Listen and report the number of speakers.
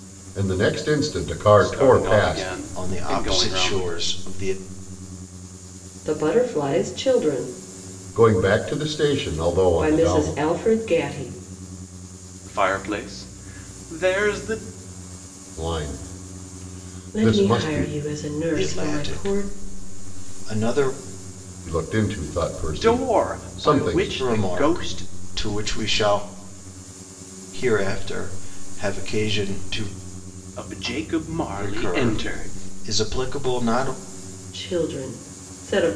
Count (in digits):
4